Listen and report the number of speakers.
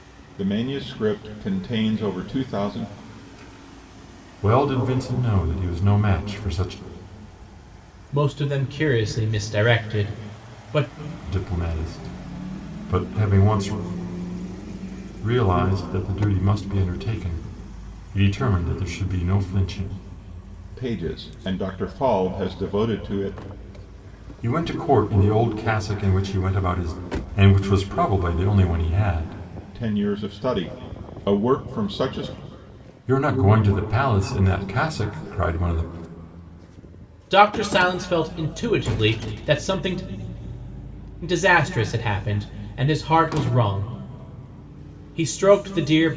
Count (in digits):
3